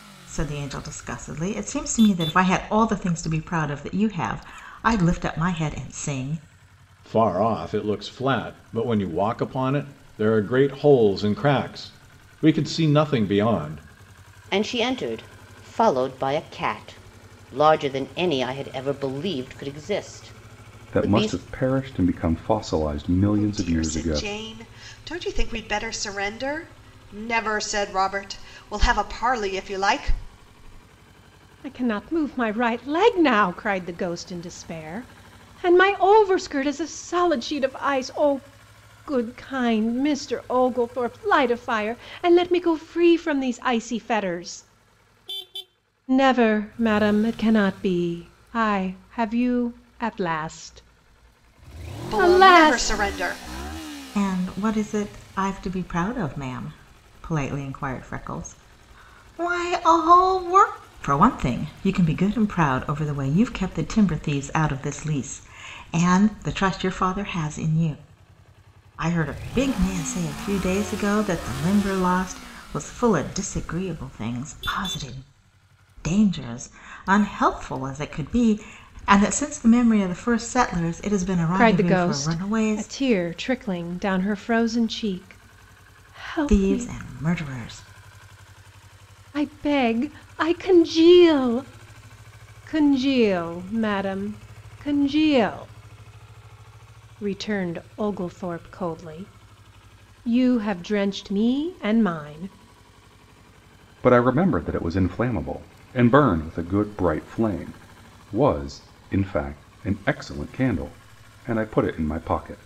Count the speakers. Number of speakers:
6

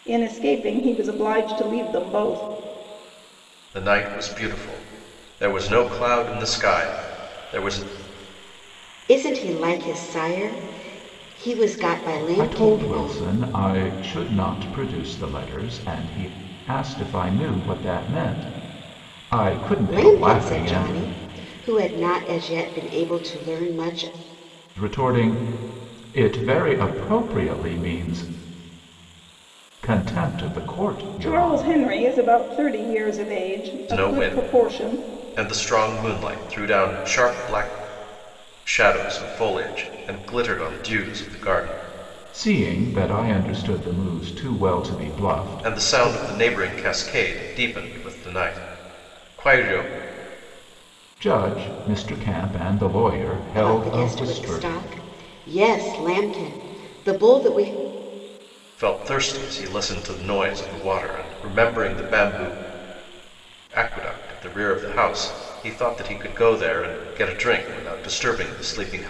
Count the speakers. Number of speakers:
4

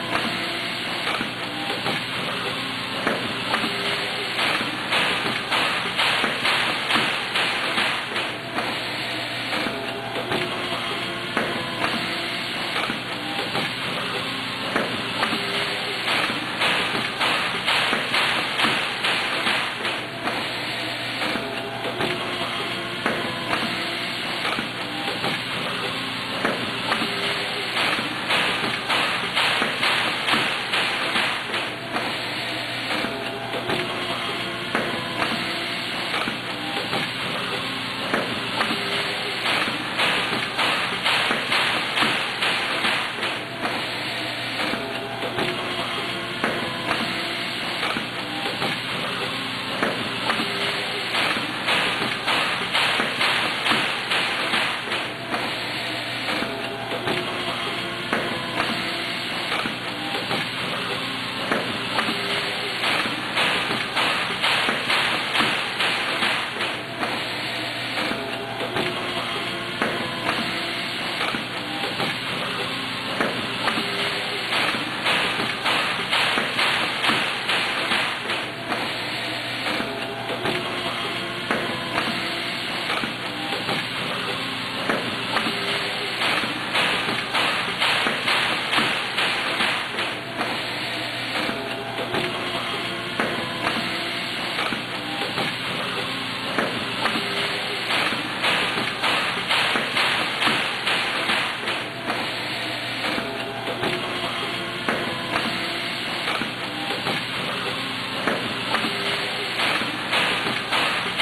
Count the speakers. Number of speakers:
0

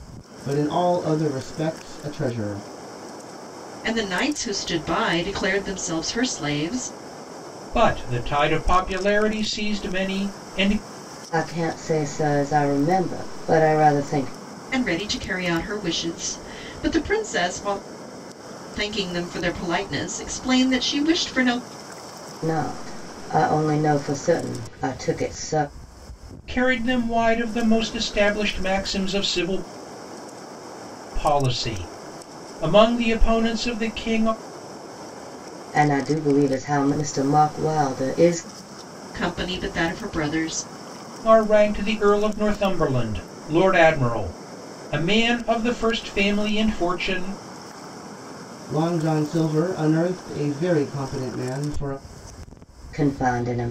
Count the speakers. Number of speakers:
4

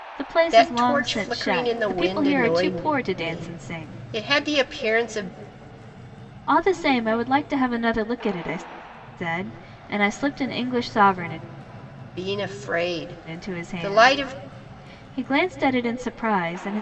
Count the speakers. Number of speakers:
2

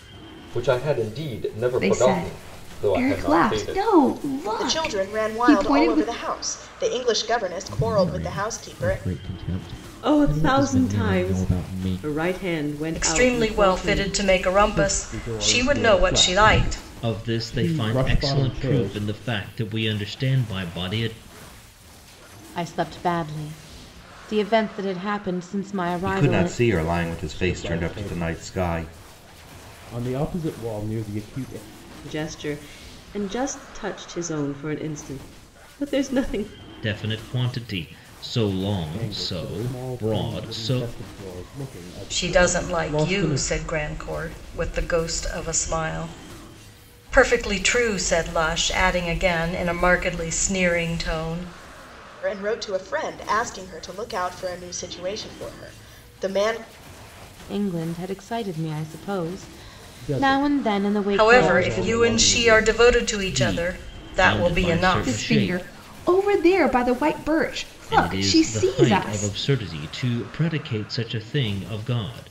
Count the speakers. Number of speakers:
10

